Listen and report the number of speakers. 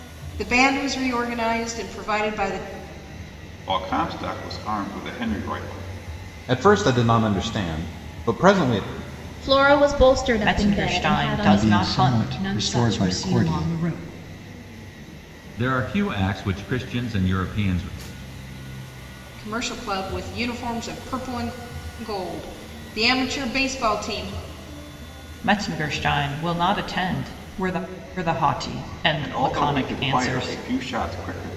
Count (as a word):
eight